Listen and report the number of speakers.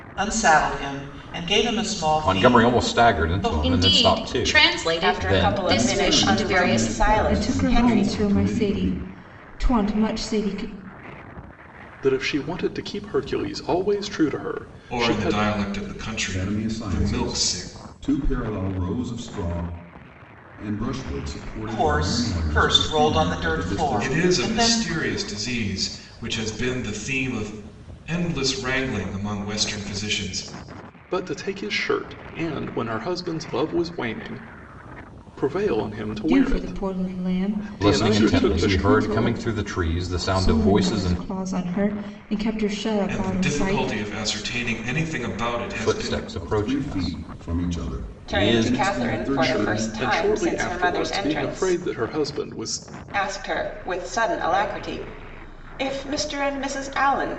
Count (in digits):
8